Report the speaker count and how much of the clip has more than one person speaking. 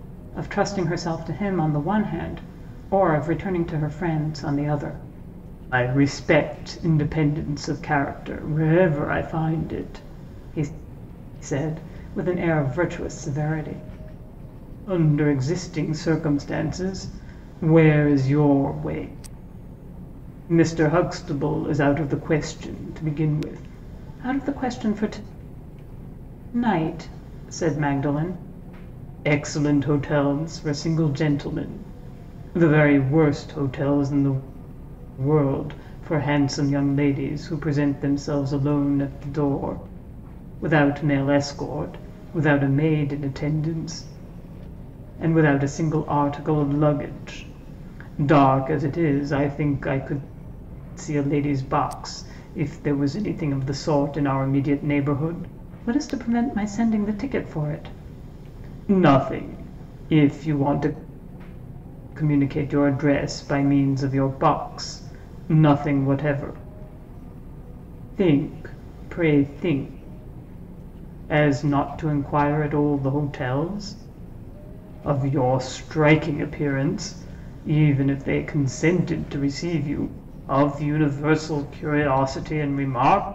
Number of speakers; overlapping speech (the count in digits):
1, no overlap